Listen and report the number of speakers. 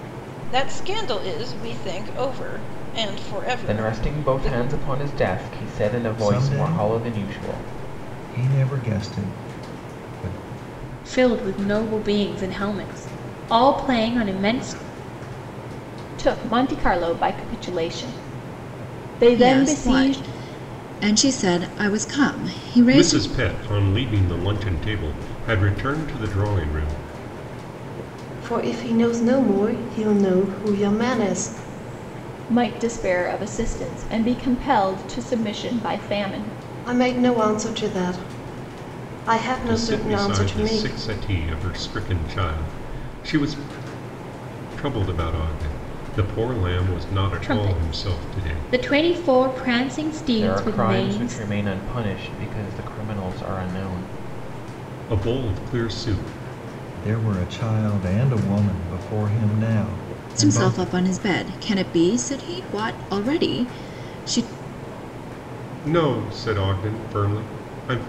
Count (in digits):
8